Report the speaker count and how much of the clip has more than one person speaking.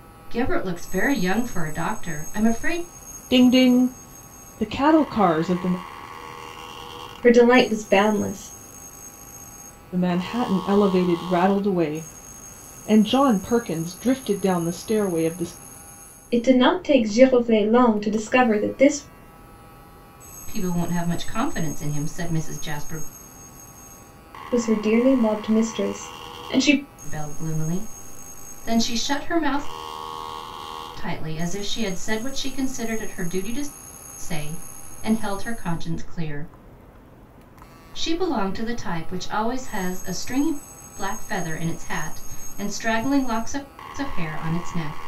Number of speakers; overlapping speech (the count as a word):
three, no overlap